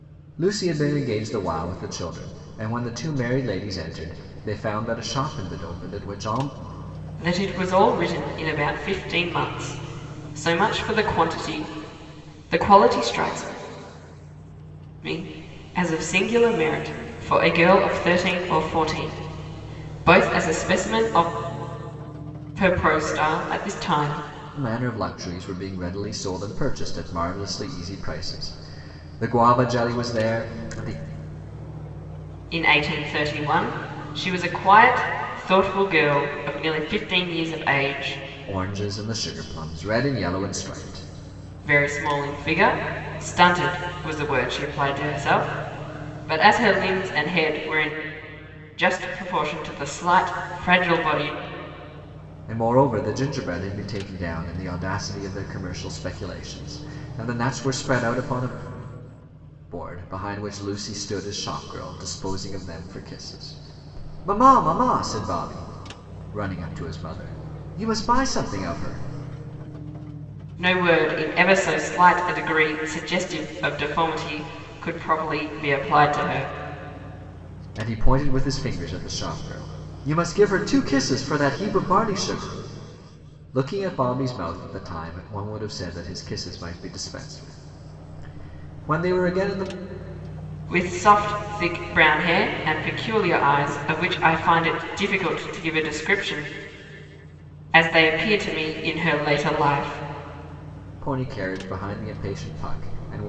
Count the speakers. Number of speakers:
two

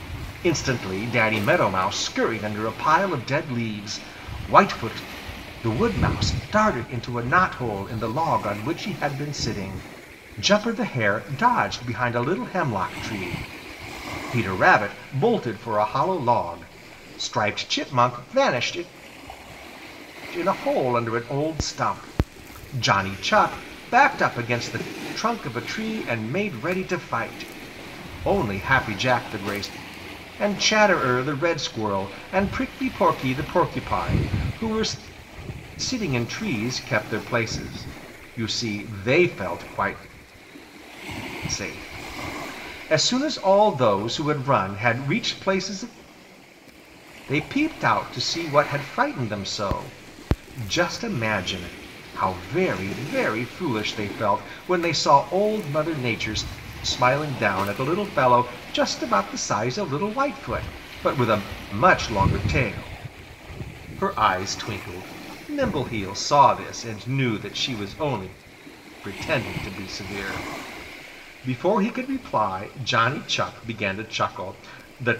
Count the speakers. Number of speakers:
one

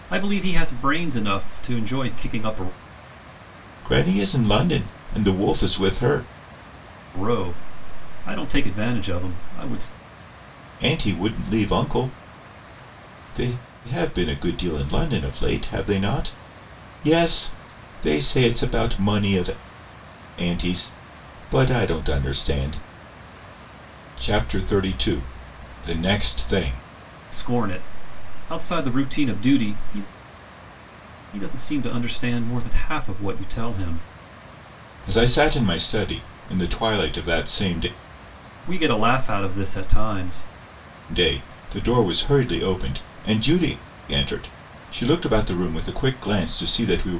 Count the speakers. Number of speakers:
two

